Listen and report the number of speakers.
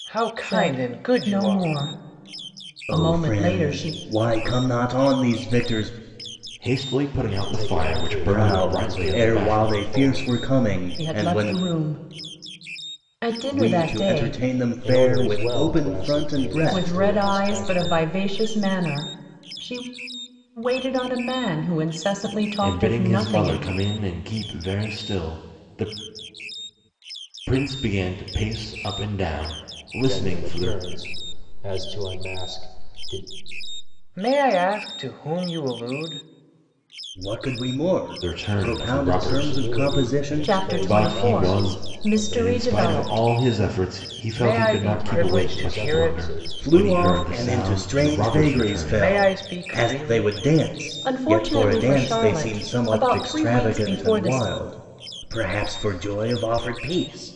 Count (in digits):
5